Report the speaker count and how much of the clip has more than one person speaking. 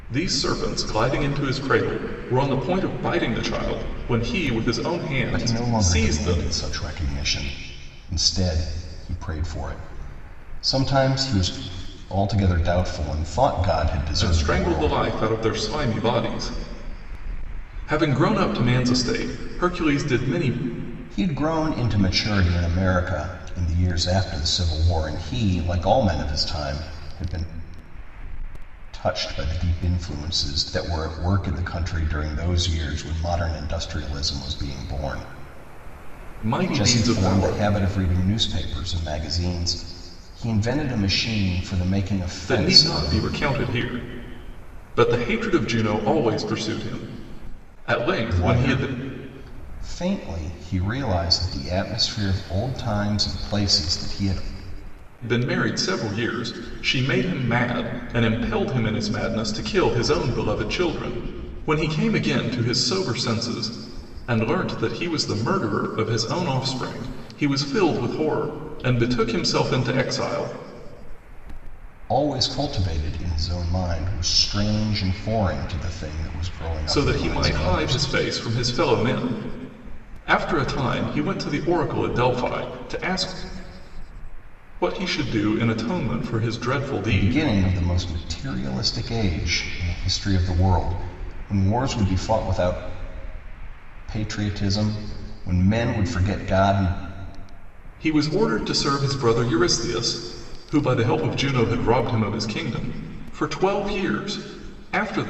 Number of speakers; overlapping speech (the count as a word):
two, about 6%